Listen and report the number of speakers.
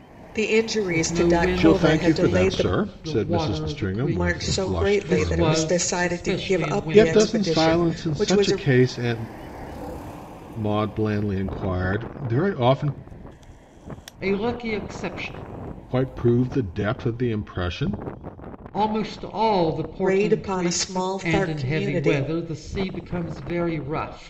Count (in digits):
3